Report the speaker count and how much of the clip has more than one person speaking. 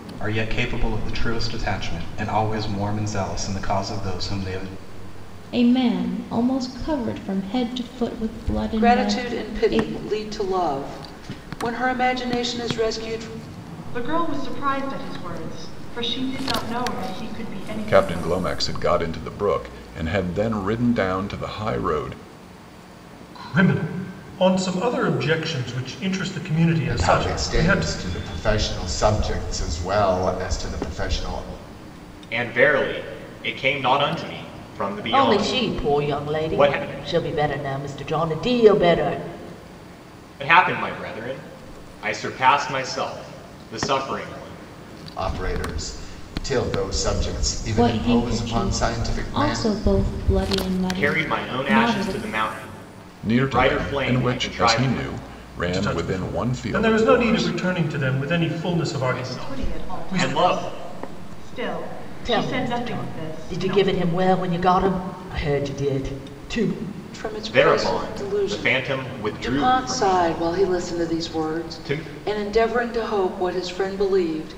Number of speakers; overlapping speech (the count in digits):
9, about 25%